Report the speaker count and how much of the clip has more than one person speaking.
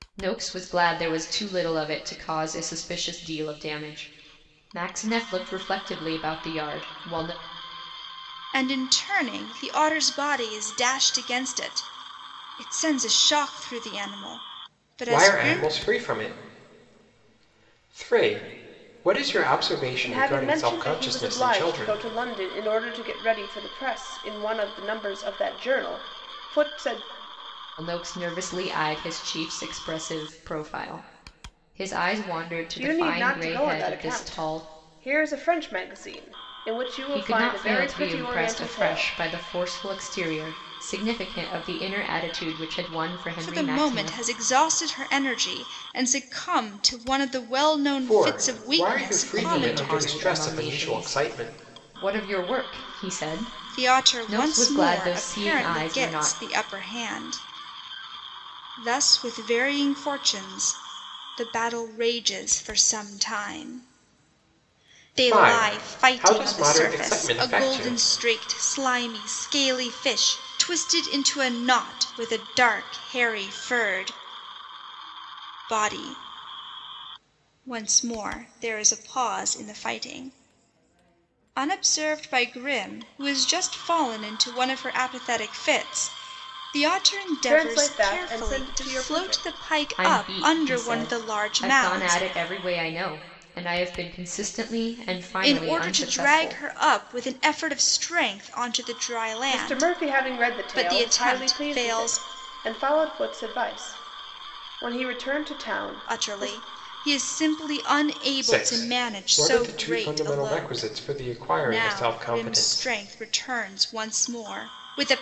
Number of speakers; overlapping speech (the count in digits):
4, about 26%